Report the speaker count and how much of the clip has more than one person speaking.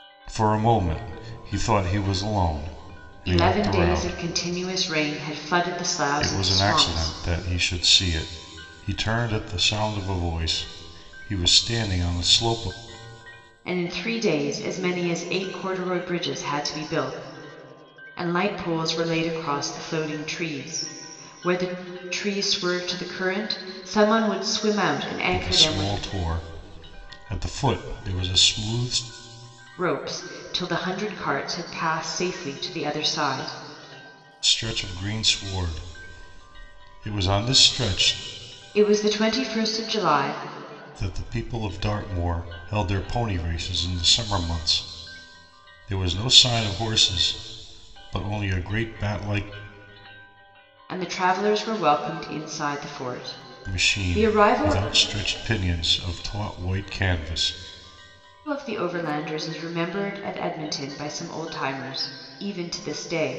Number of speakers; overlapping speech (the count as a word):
two, about 6%